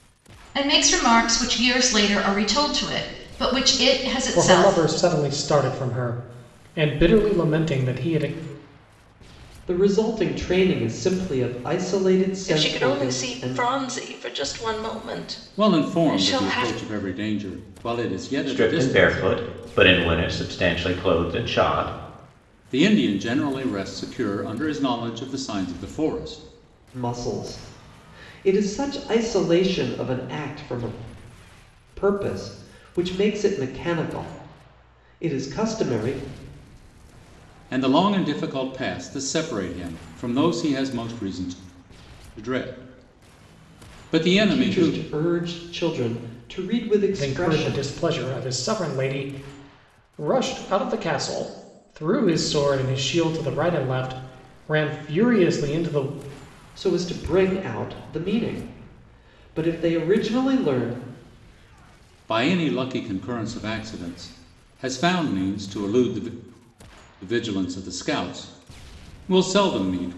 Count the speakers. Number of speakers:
6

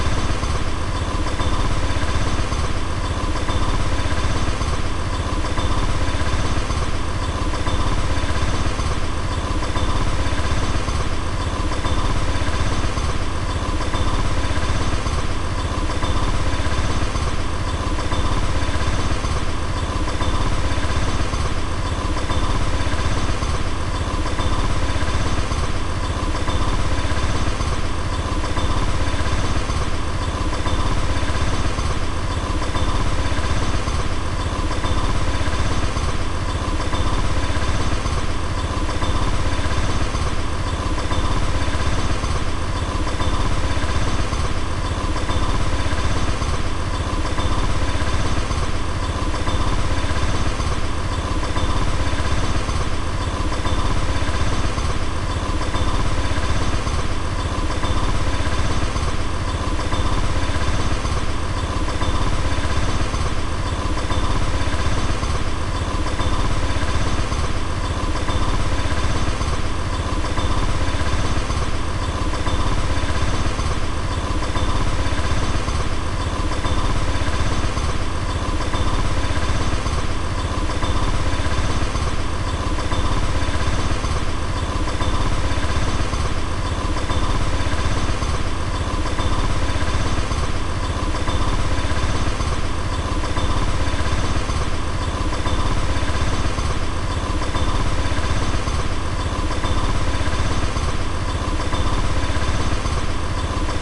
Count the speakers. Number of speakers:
0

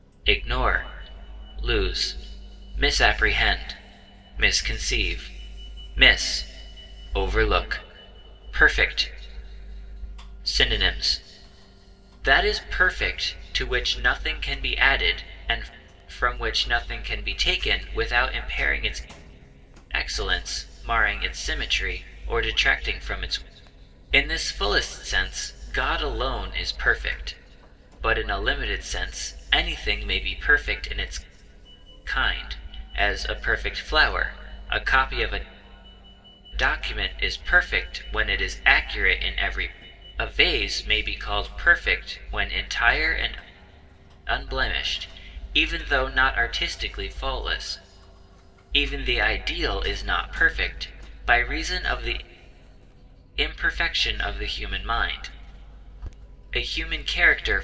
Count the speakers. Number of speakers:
1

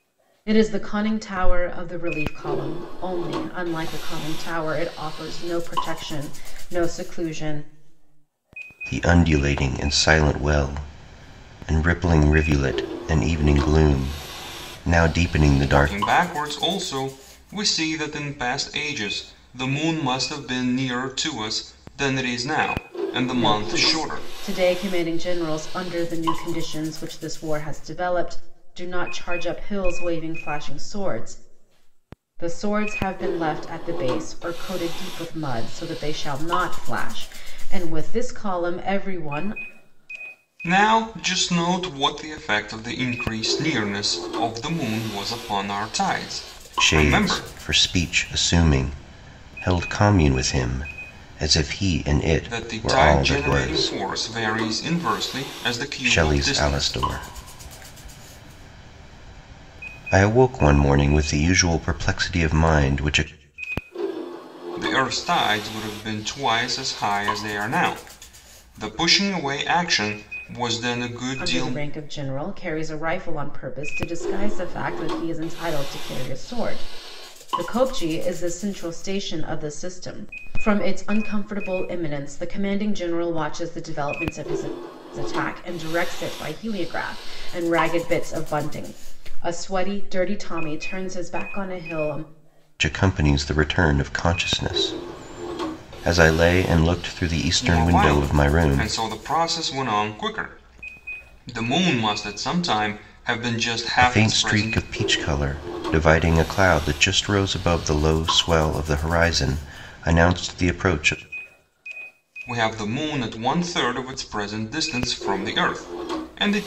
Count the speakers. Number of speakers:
3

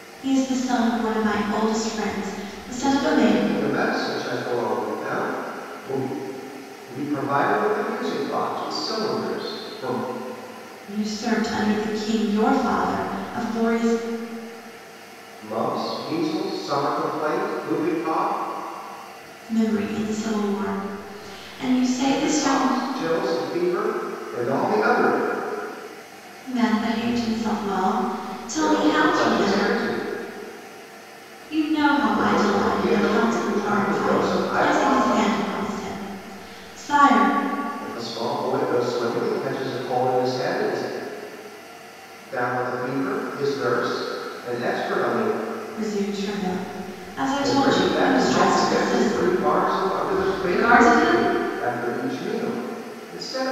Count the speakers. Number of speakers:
2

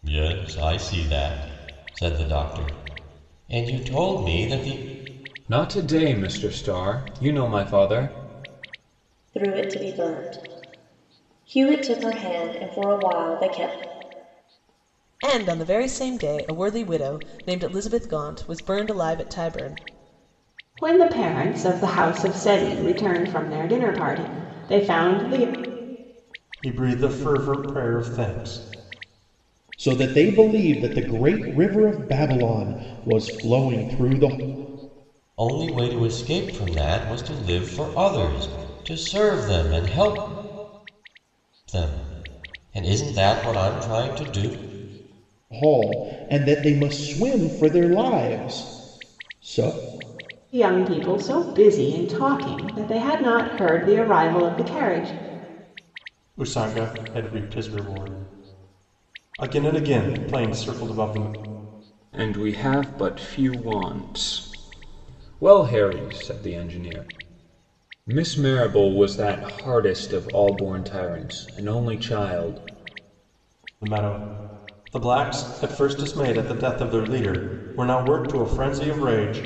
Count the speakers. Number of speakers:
7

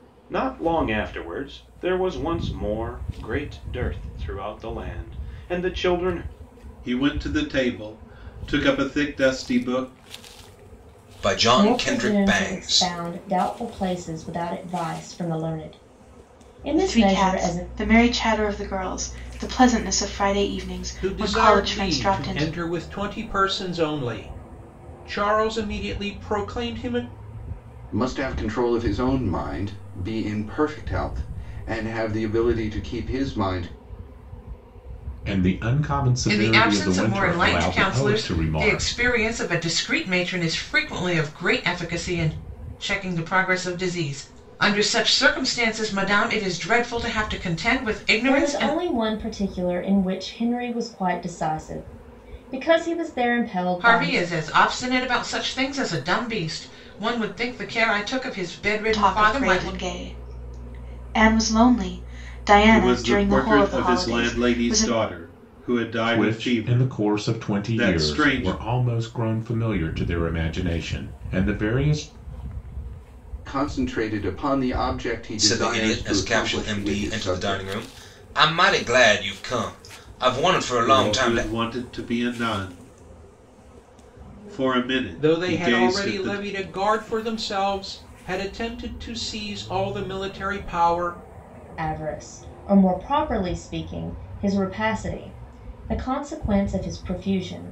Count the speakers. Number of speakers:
9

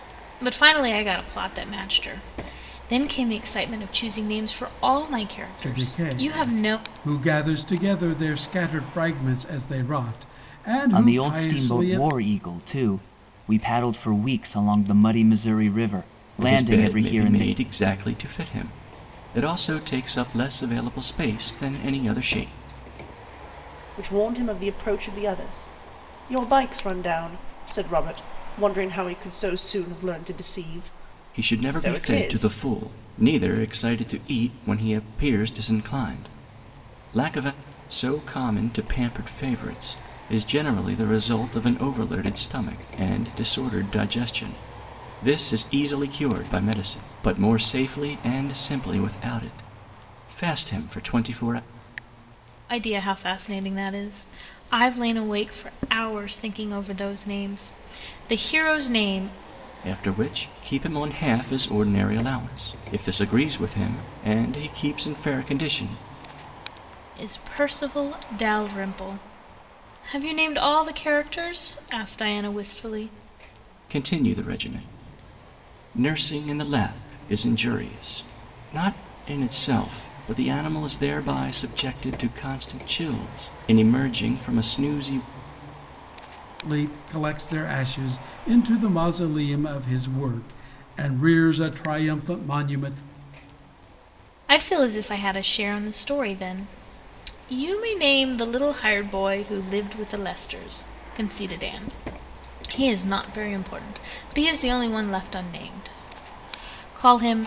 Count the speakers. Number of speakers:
5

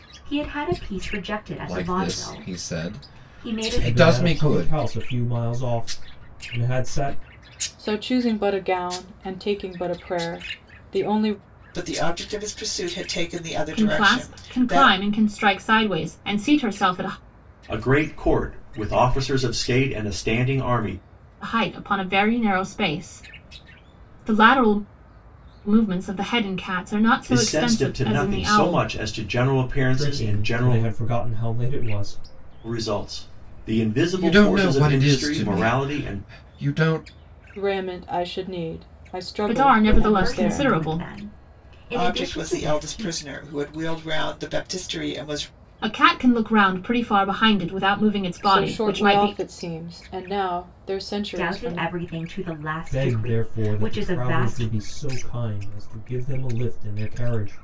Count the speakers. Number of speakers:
7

